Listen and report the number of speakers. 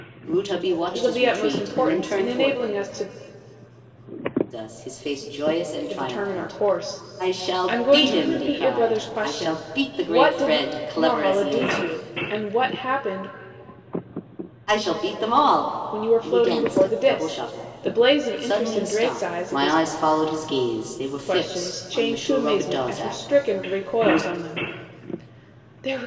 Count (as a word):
two